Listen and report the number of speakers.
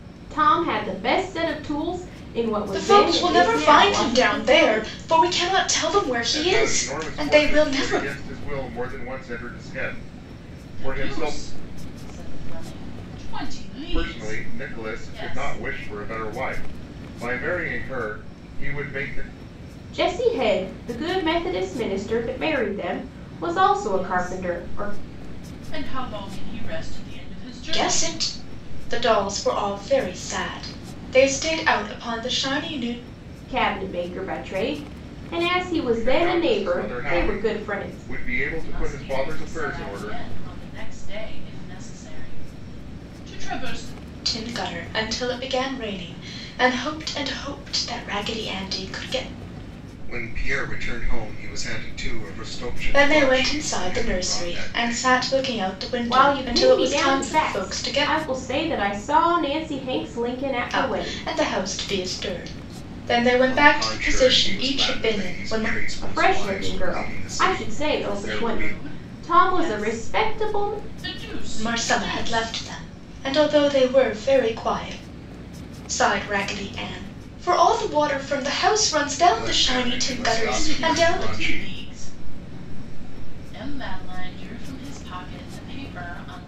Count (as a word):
four